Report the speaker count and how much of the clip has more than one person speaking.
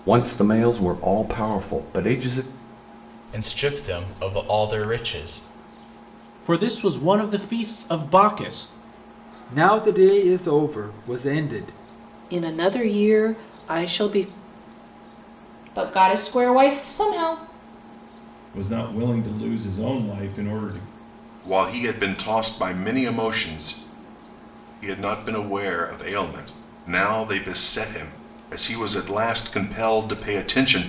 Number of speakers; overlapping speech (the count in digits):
8, no overlap